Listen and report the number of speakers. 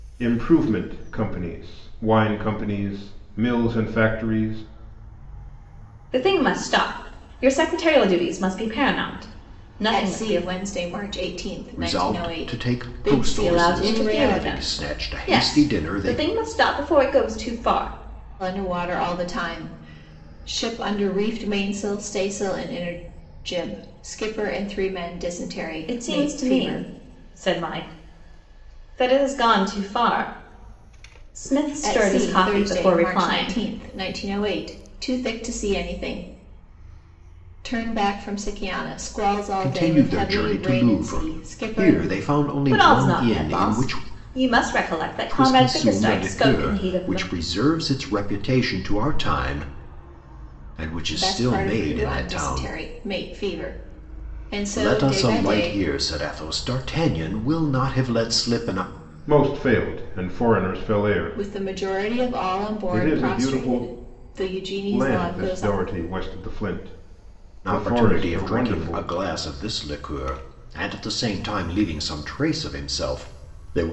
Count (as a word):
four